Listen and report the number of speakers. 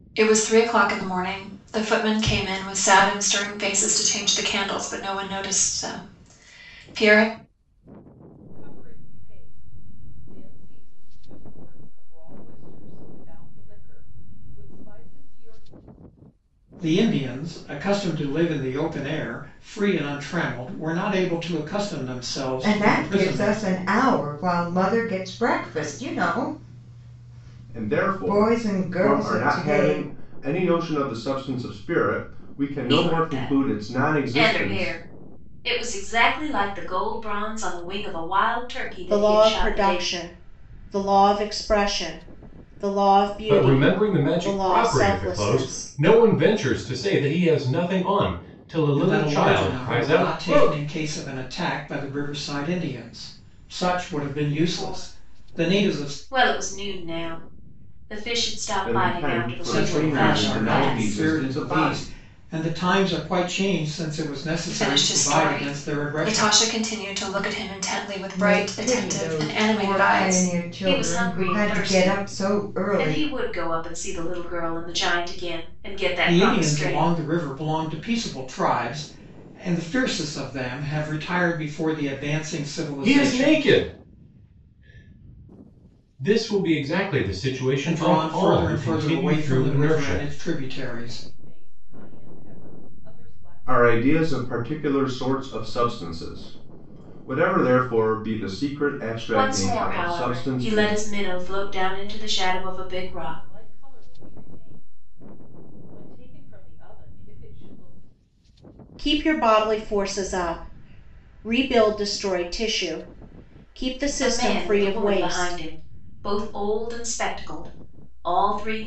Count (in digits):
8